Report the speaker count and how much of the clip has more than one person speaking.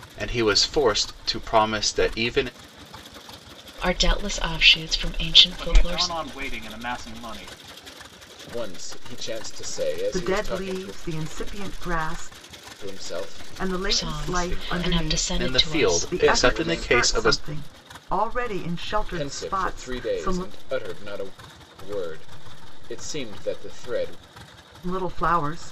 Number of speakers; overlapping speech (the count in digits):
5, about 26%